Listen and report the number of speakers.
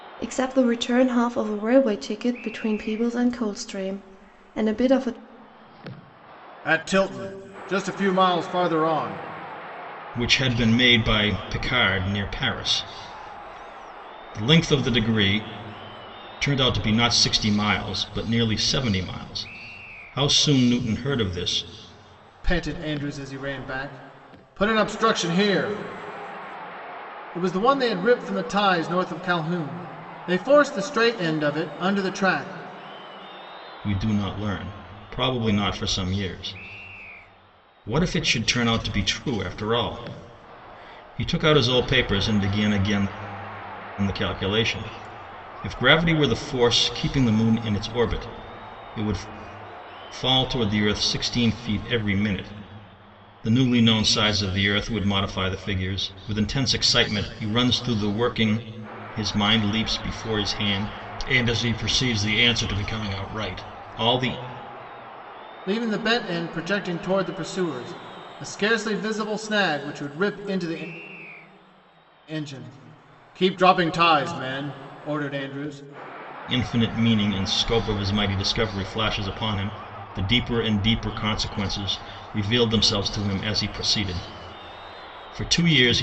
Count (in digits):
3